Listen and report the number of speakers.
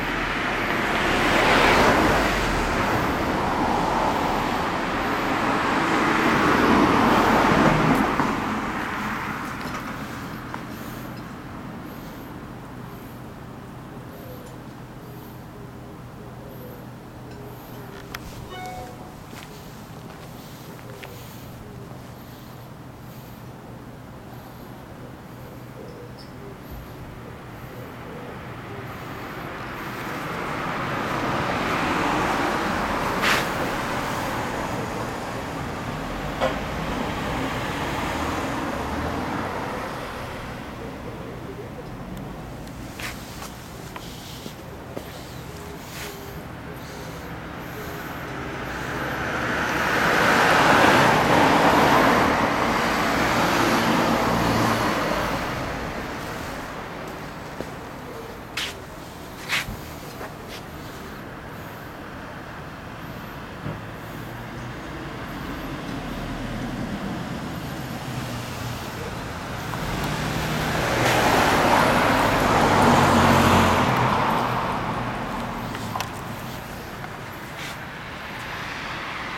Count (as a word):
zero